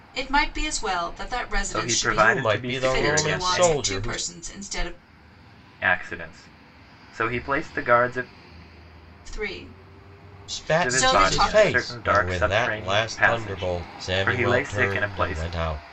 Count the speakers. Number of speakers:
3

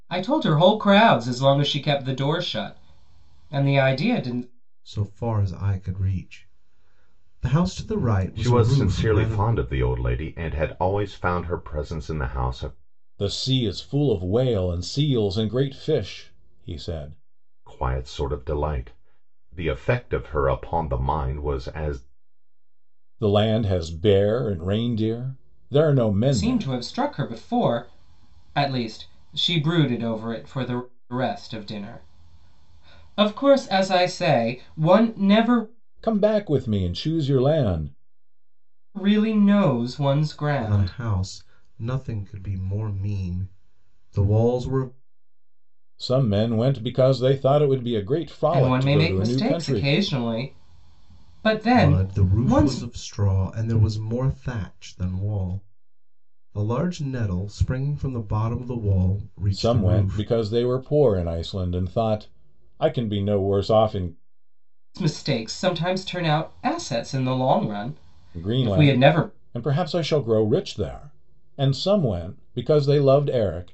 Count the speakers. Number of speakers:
4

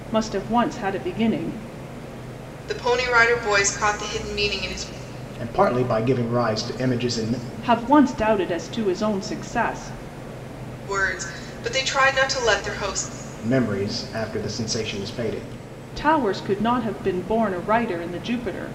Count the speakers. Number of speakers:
3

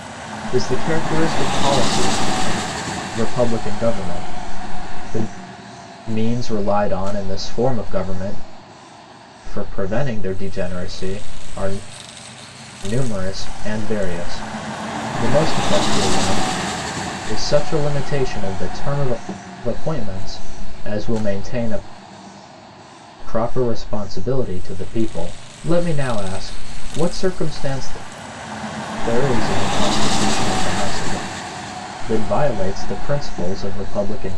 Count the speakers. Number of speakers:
1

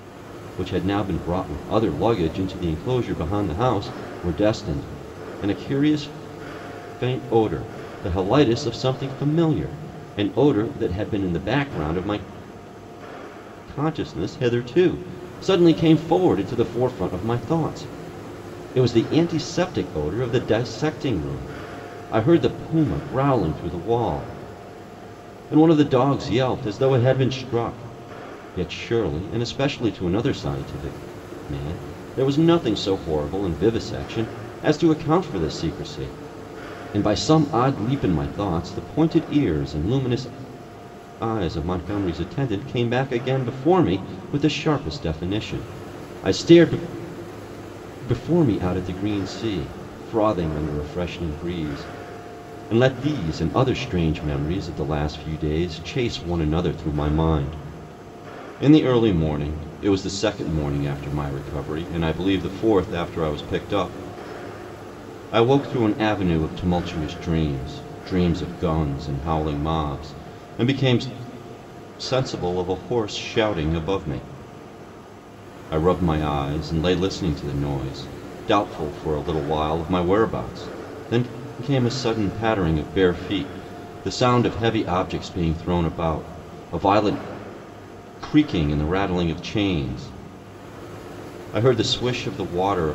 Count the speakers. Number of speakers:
1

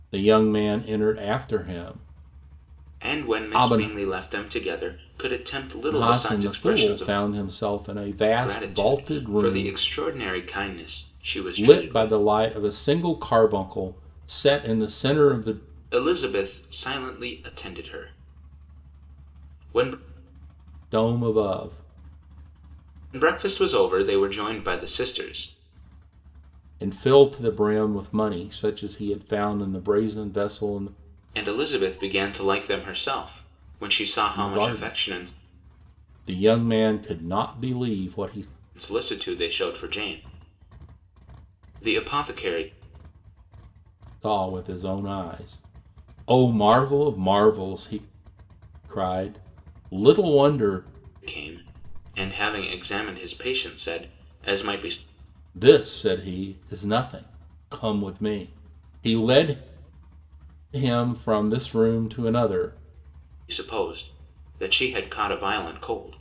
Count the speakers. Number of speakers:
2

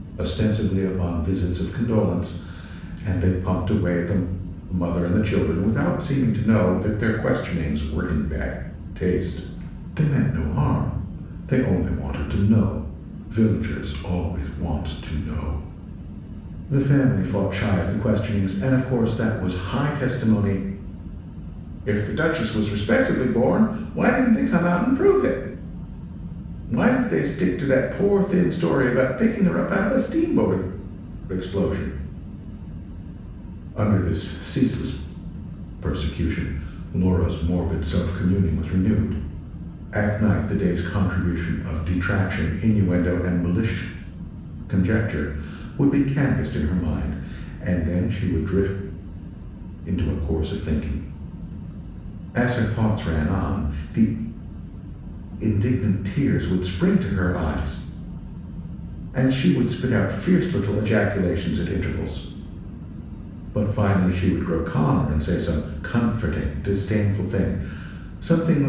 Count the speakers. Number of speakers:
1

